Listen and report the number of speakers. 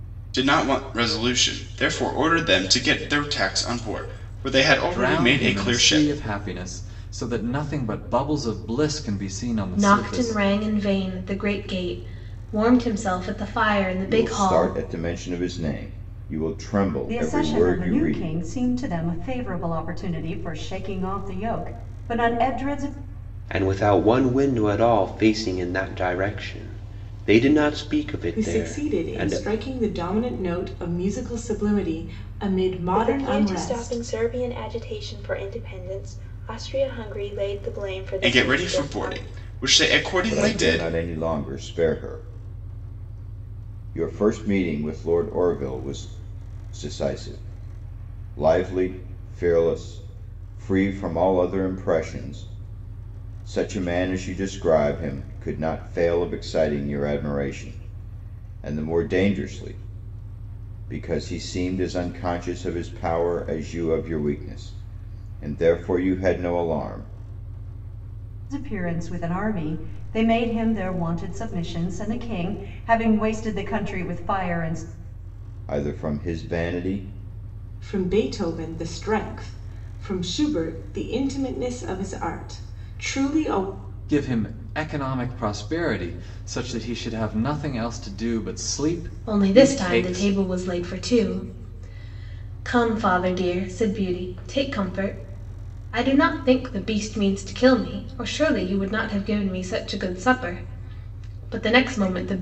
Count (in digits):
8